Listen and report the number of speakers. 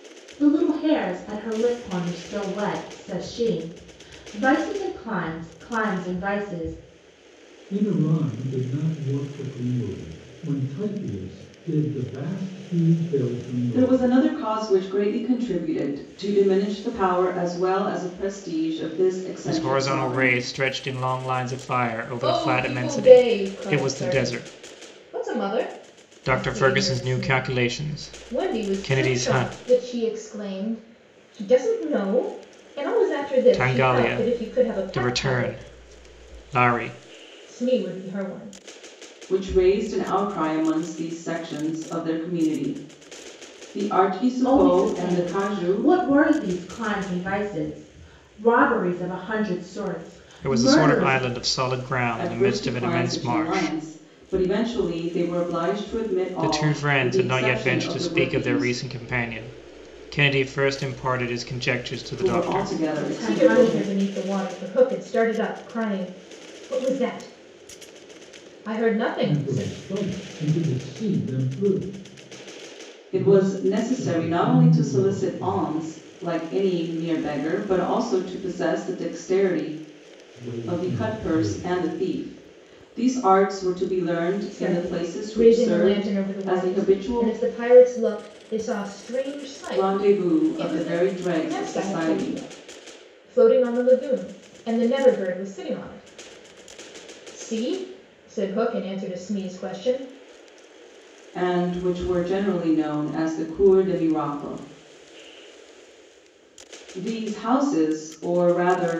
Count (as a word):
five